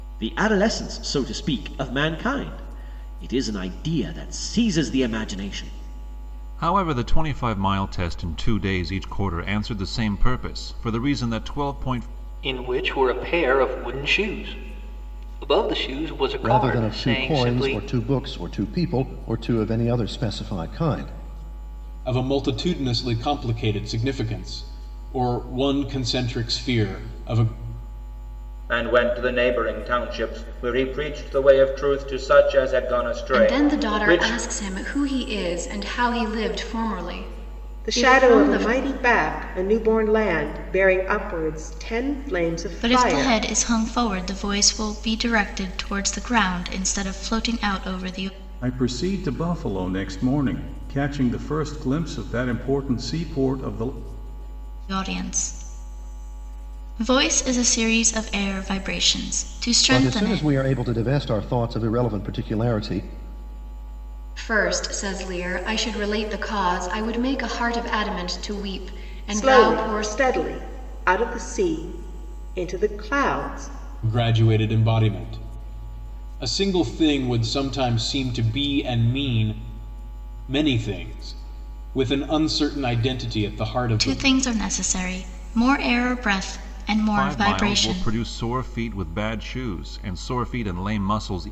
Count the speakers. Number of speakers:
ten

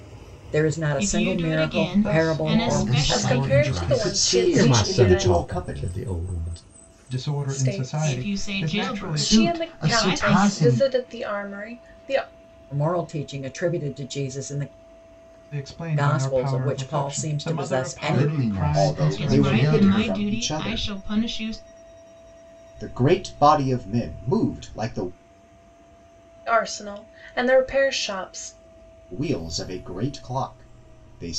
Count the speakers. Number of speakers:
seven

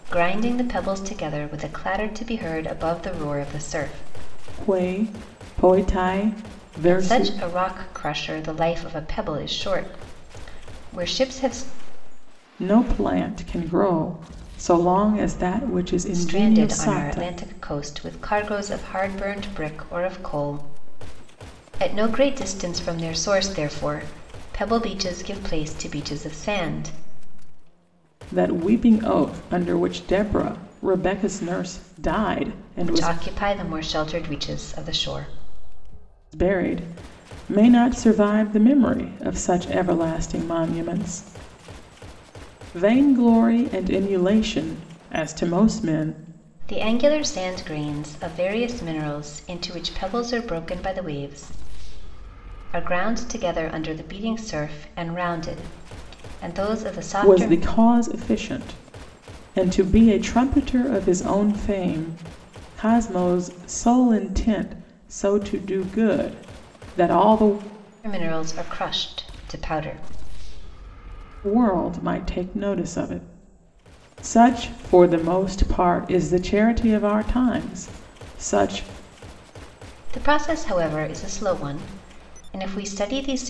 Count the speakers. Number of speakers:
two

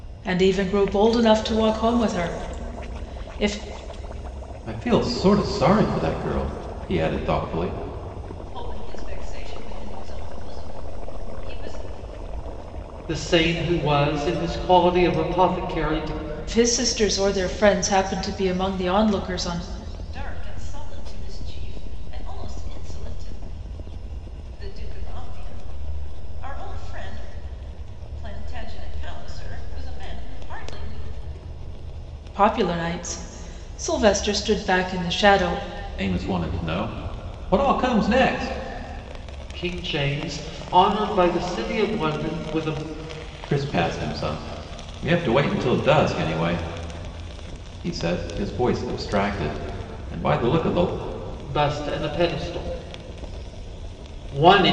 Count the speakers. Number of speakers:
four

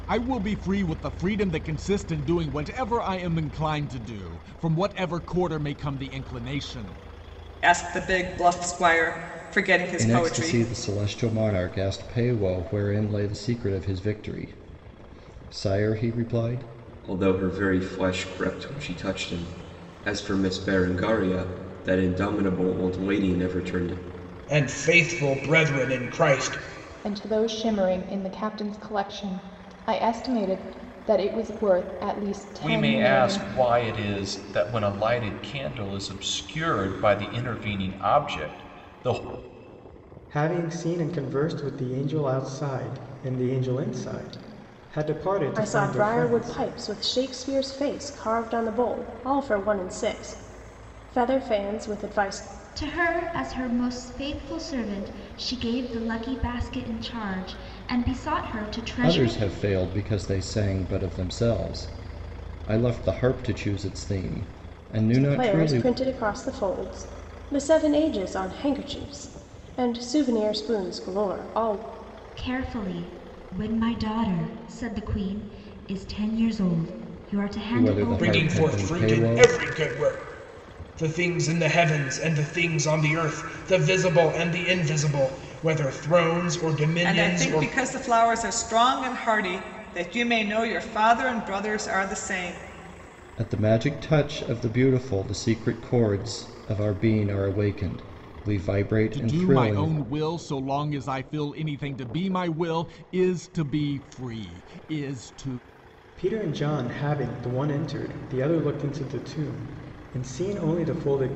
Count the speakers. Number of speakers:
ten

